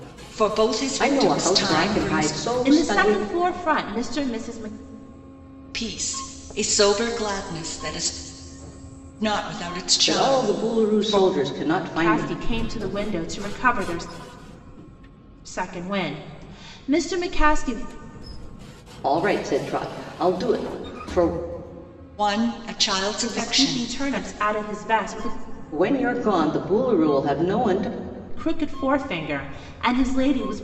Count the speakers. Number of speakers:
three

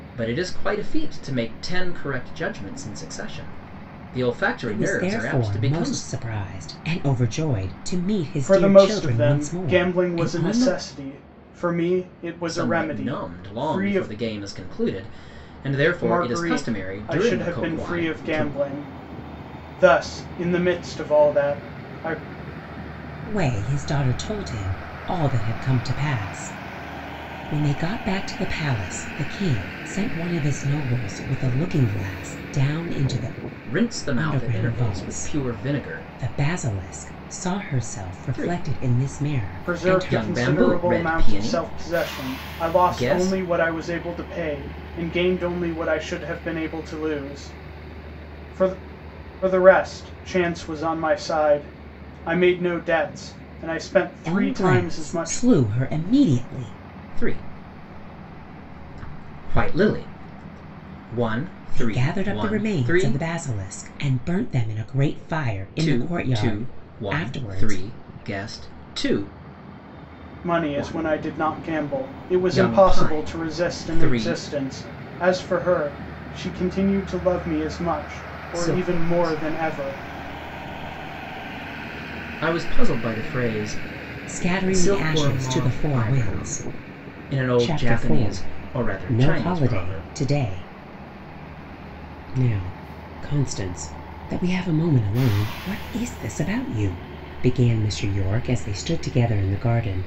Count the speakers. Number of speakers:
three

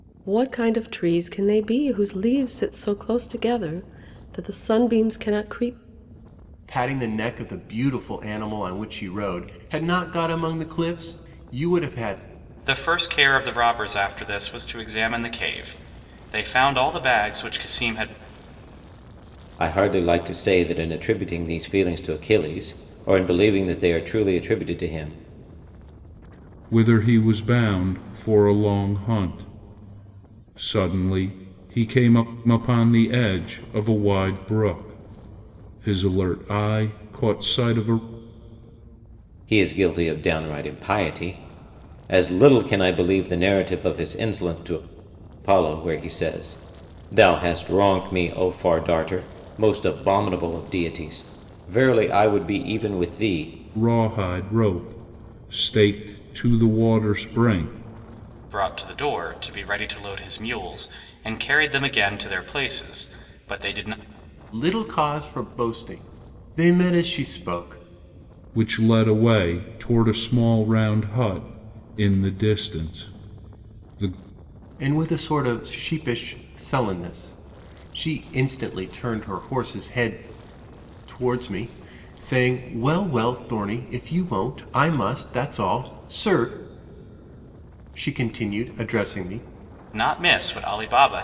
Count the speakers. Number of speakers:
five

